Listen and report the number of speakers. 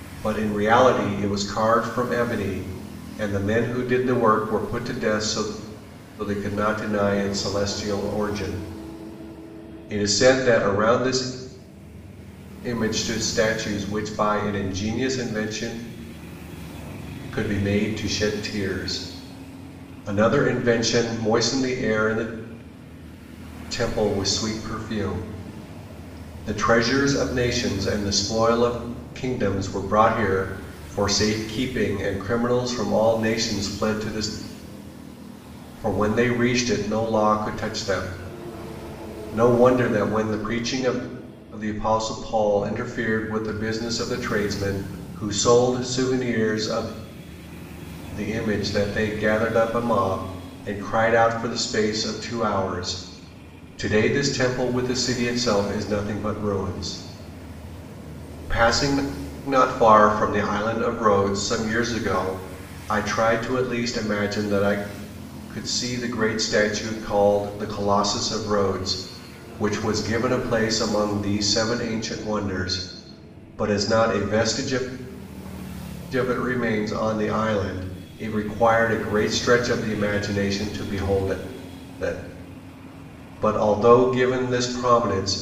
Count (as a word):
one